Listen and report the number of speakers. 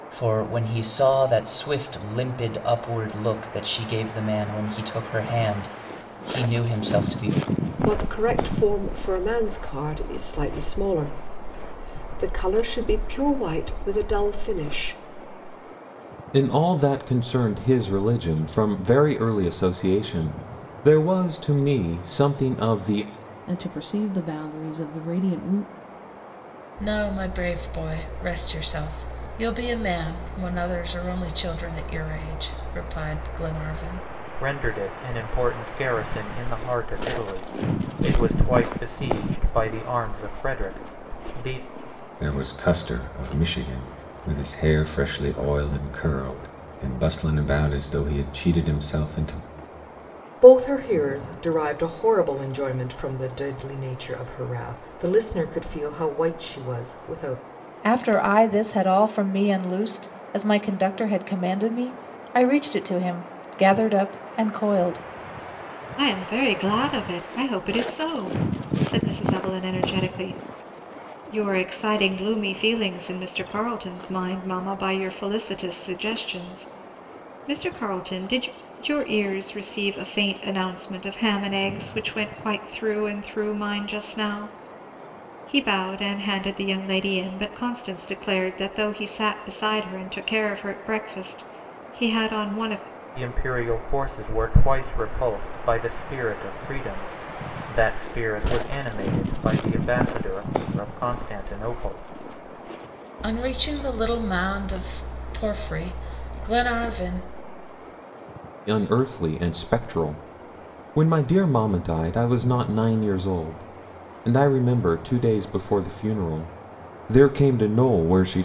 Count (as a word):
ten